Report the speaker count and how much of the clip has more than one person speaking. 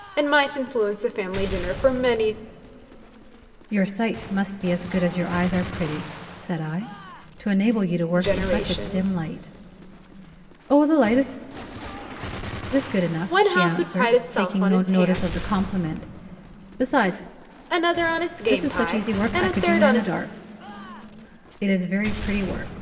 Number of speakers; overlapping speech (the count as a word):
two, about 20%